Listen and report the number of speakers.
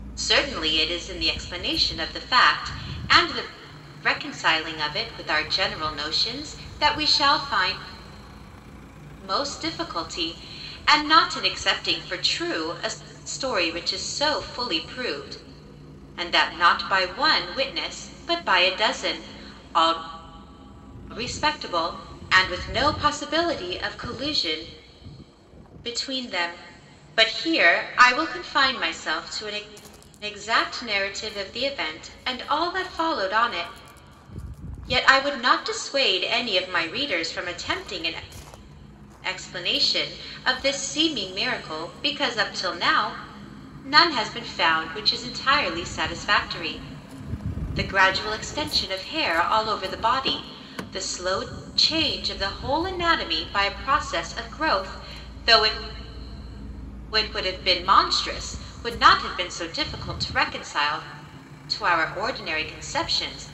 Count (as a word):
one